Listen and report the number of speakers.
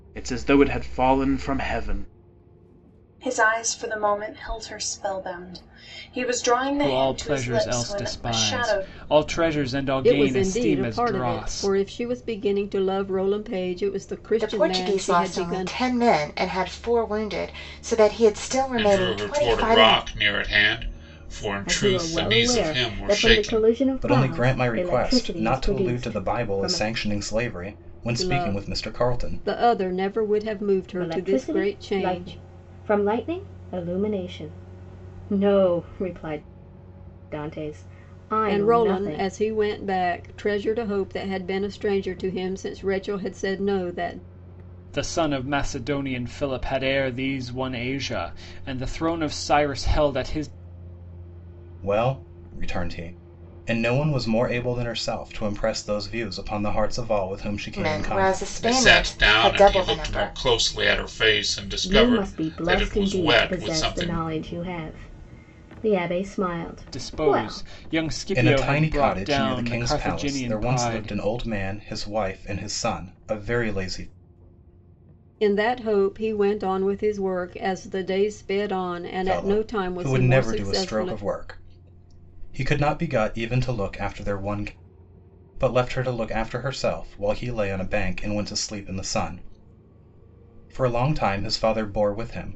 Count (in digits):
8